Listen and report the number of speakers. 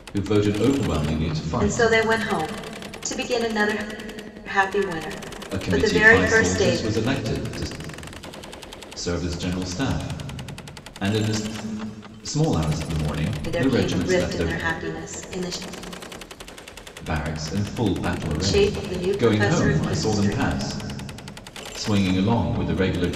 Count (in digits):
2